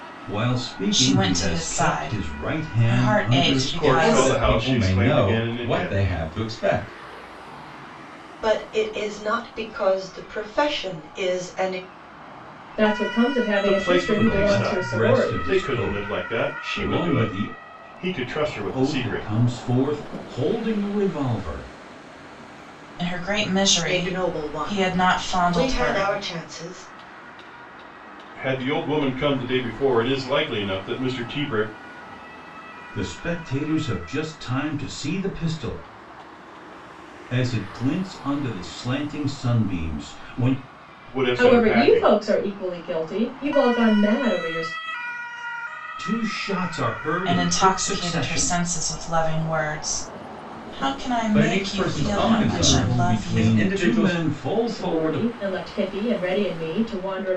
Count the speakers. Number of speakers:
6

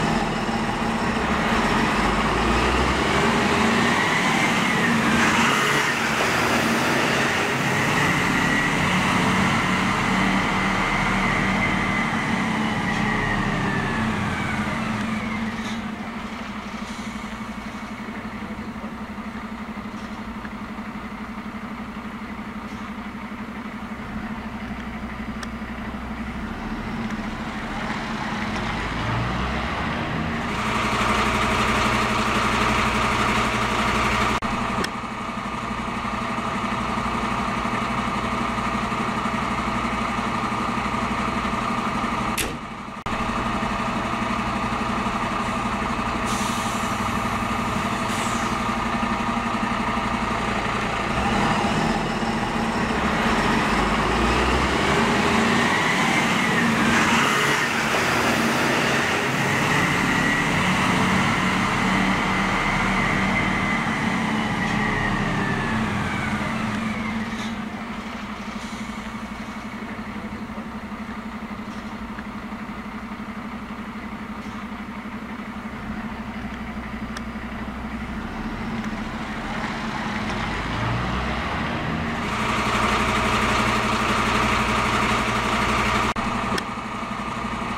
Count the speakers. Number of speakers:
0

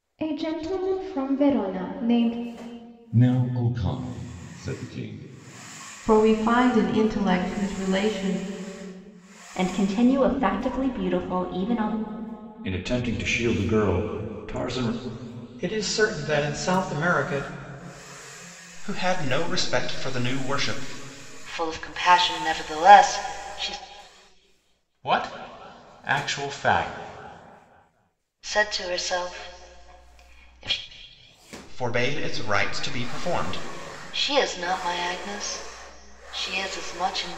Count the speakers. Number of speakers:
9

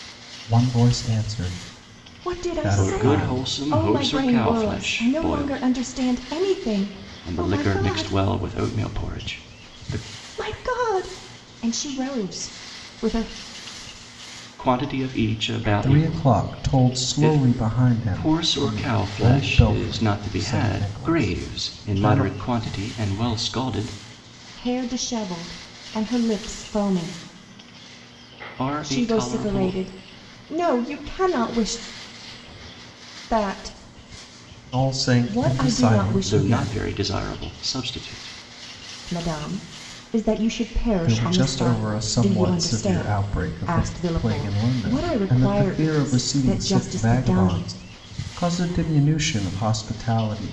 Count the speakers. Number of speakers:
3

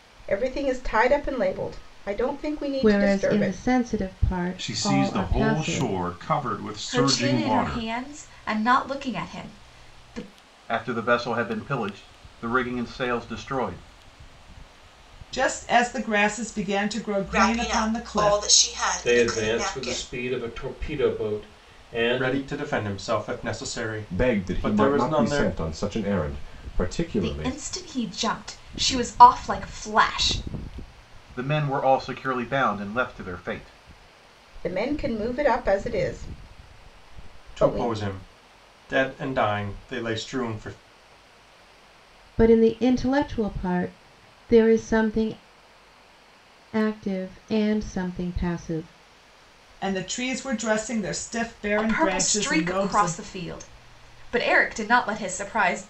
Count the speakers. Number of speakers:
10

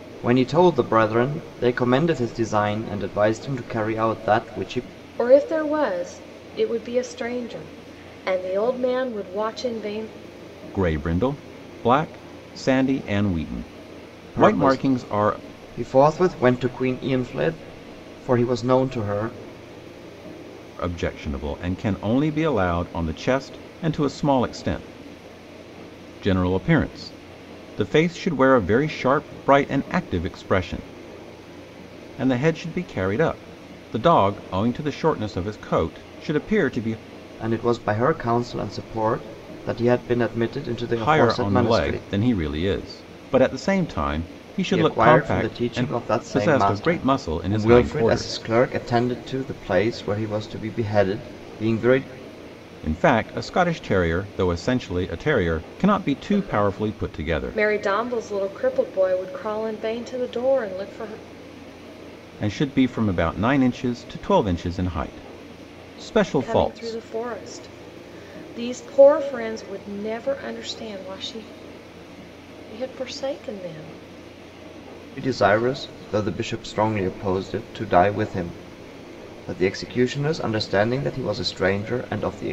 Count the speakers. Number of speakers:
3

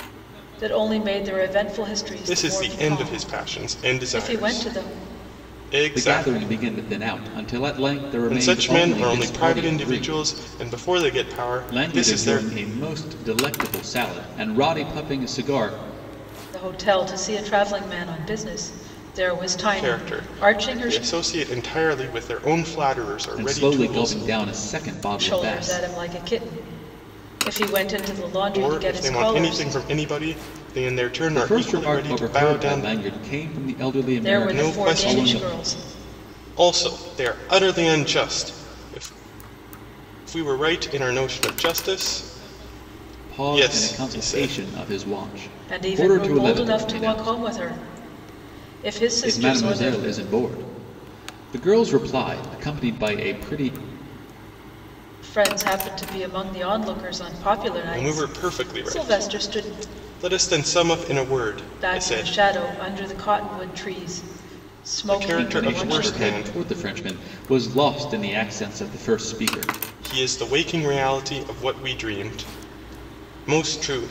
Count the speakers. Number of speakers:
3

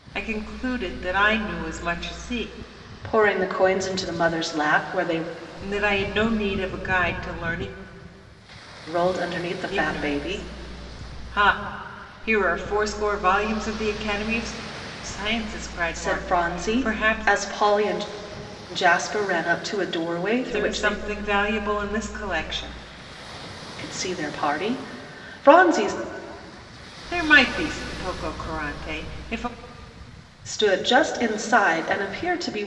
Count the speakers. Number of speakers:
2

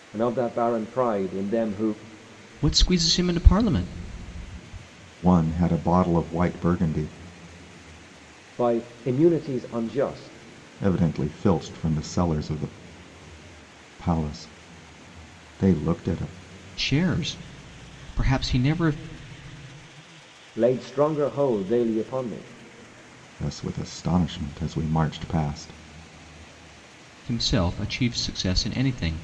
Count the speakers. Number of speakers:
3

